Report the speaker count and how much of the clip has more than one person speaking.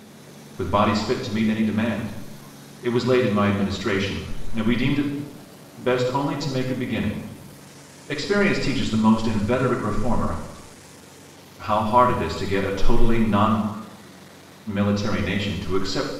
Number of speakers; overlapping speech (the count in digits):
1, no overlap